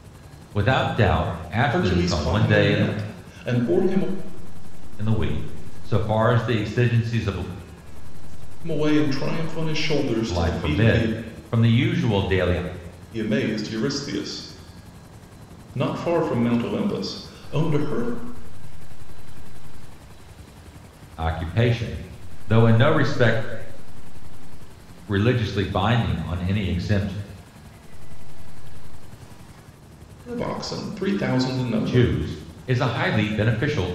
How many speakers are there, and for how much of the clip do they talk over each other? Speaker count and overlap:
3, about 21%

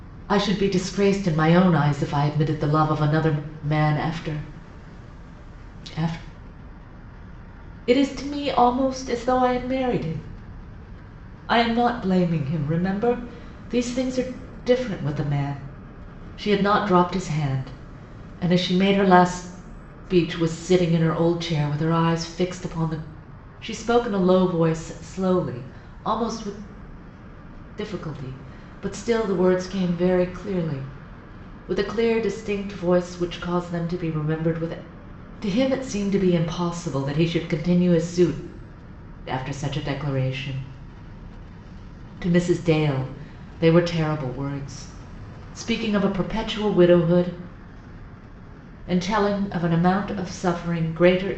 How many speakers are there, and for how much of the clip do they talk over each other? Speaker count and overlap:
1, no overlap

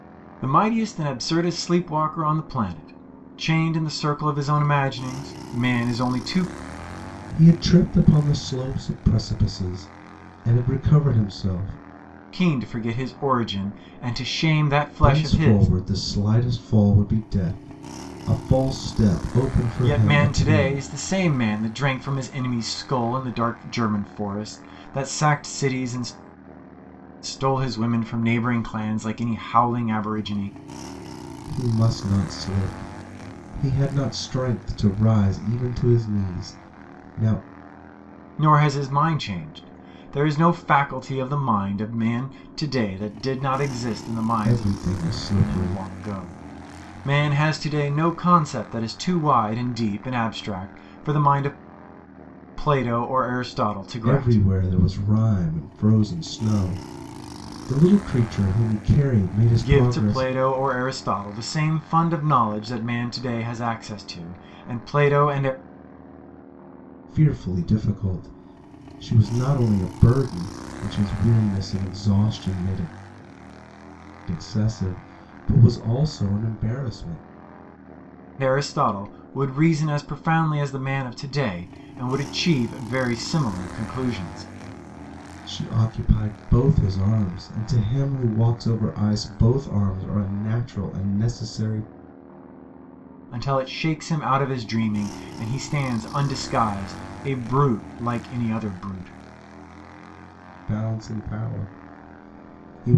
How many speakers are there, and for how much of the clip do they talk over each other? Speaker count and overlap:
2, about 4%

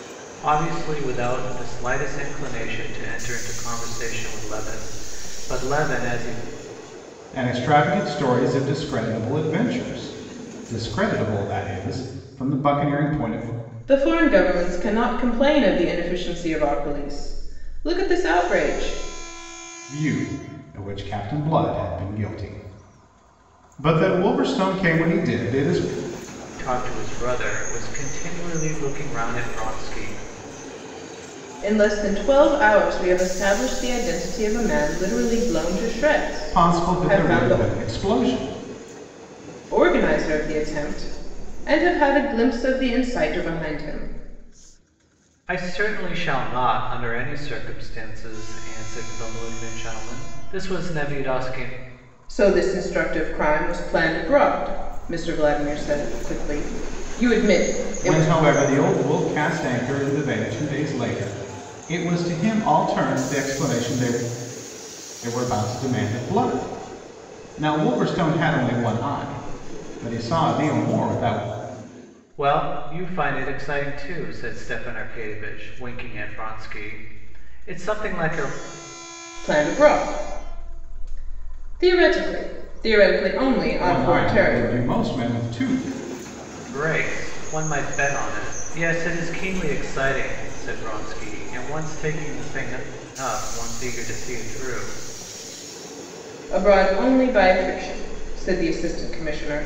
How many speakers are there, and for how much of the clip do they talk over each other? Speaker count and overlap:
3, about 3%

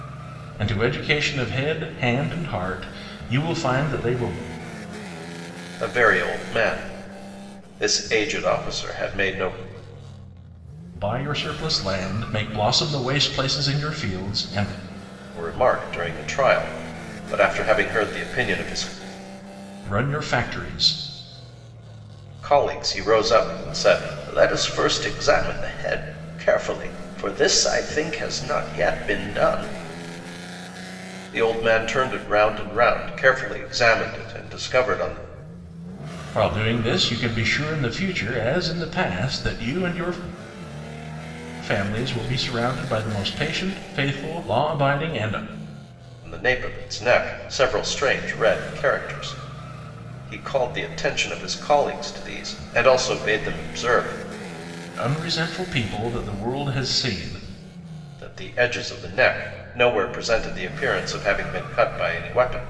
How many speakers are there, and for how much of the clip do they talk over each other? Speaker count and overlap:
2, no overlap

